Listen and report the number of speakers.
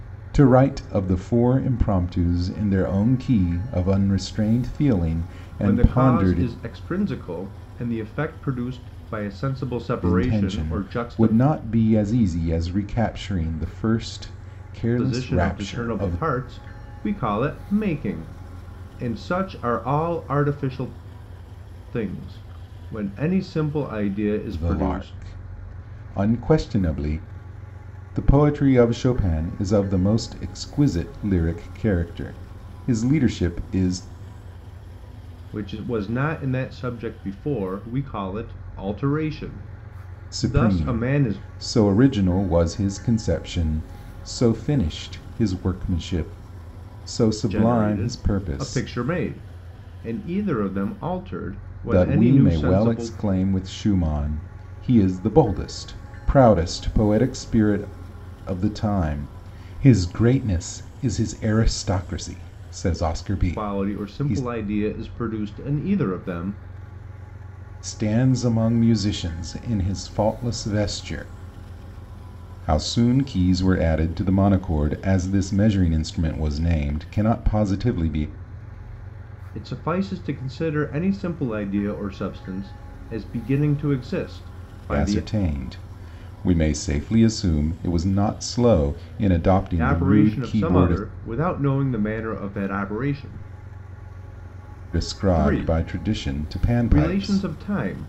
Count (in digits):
2